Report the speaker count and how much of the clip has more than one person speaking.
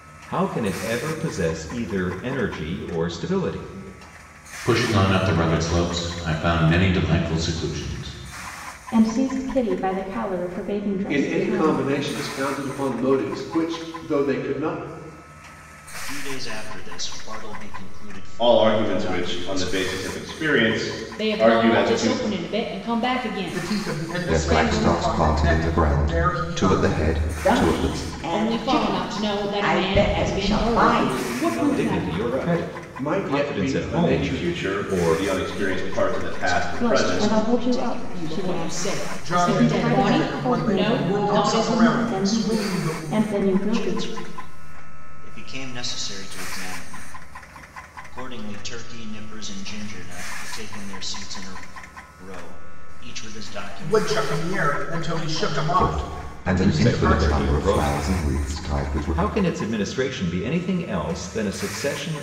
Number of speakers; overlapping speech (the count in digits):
10, about 45%